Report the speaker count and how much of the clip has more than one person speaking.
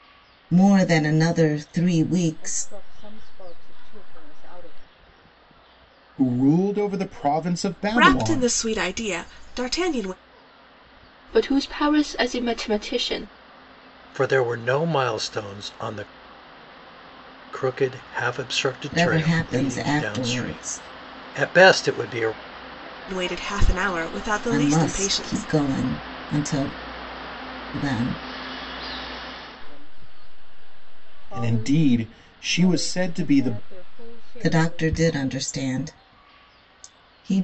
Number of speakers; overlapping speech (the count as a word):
six, about 17%